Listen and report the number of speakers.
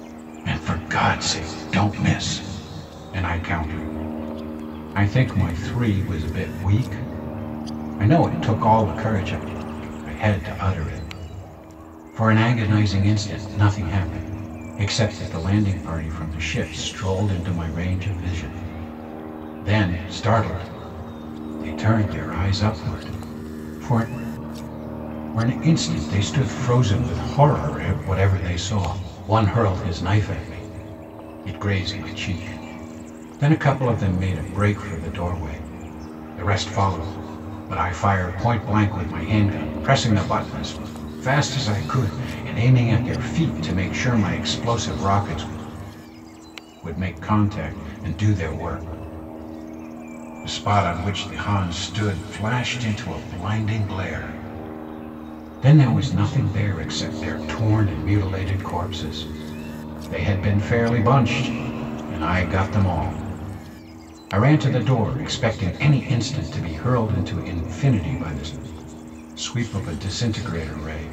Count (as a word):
one